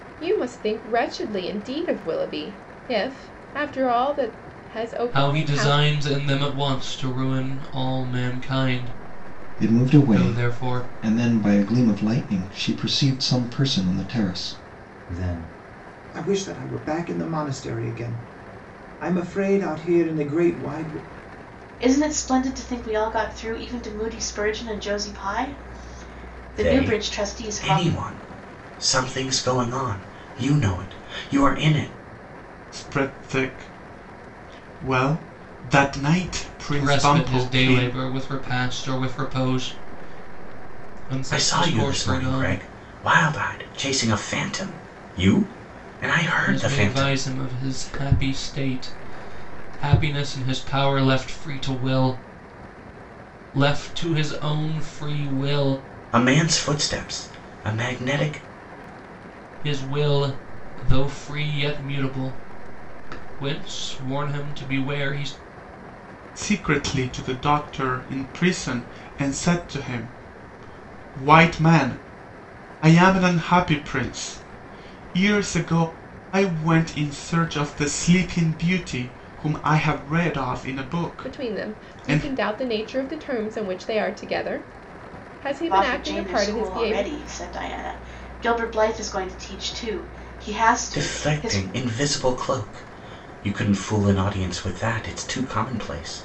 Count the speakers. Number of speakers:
seven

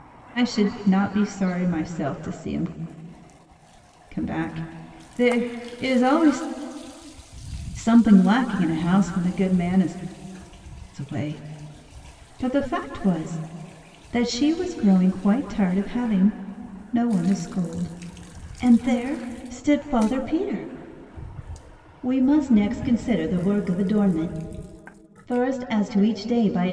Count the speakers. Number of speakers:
one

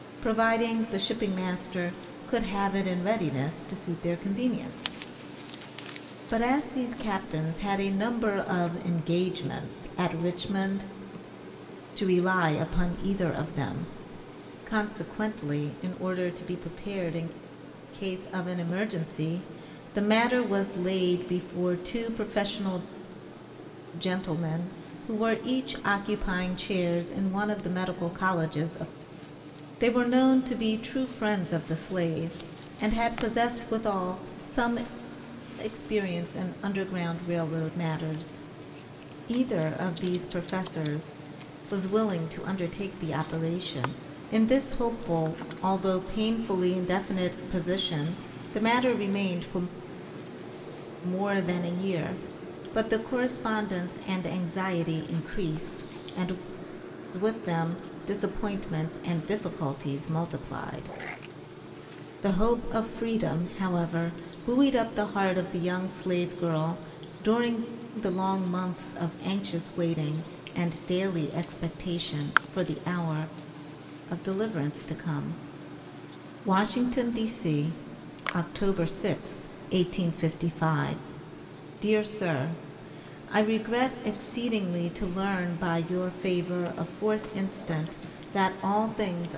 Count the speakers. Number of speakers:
one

